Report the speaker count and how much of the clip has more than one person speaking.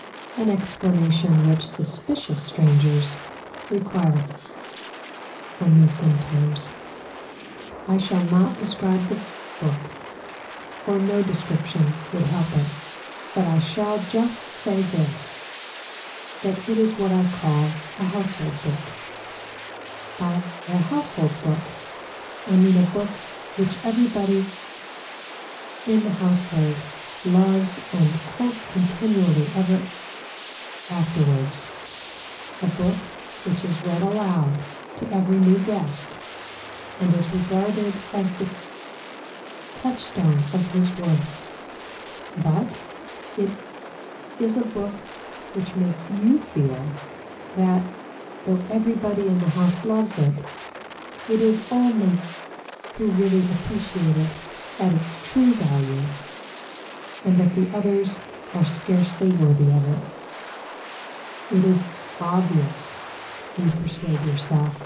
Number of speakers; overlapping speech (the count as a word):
one, no overlap